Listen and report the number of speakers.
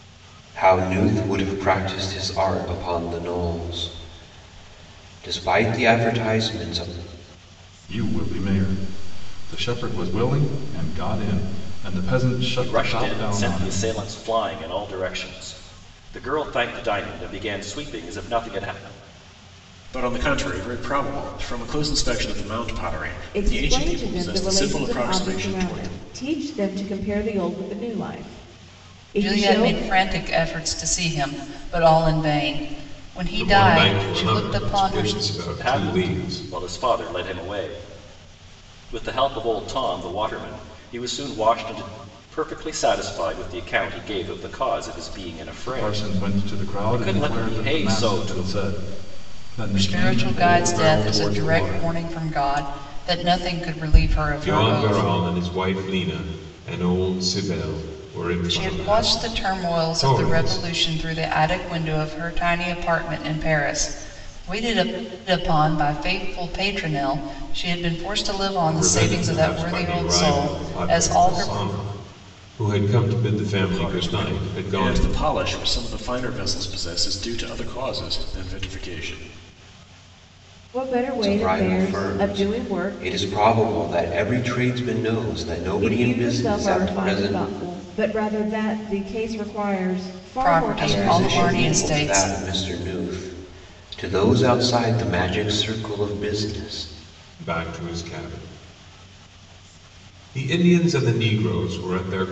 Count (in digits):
7